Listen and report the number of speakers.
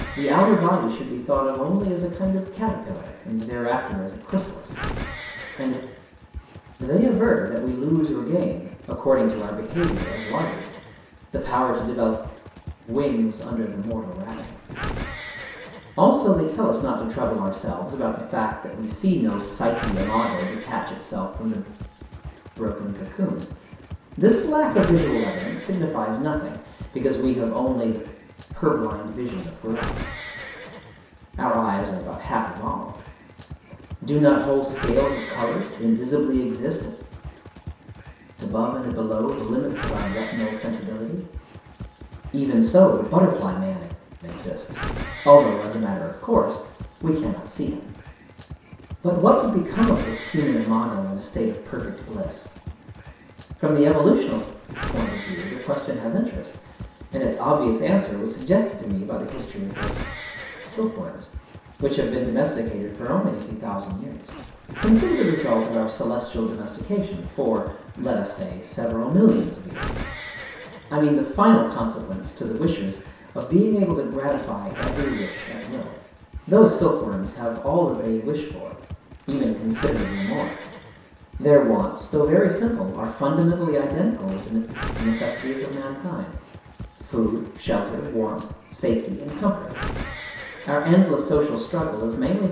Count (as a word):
one